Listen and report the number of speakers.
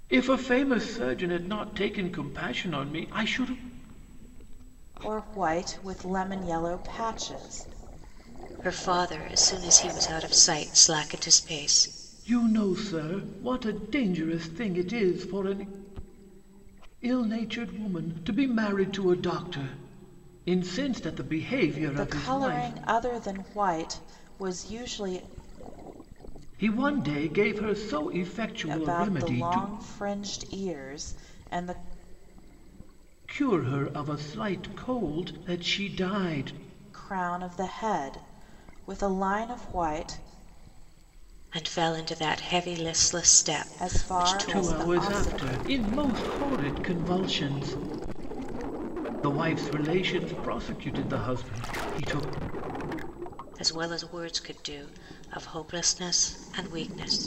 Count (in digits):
3